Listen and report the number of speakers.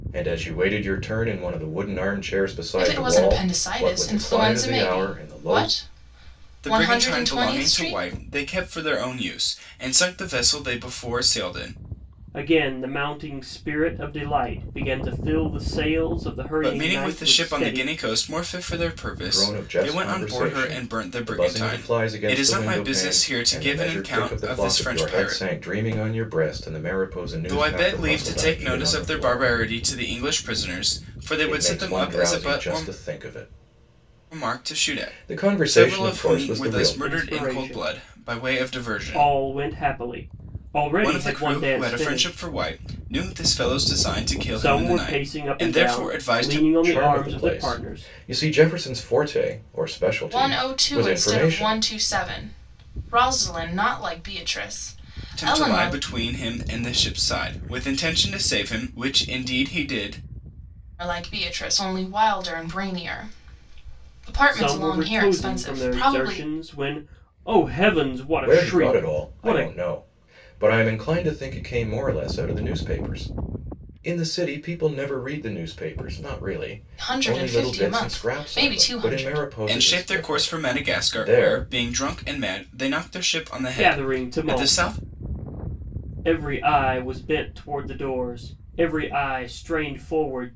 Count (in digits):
4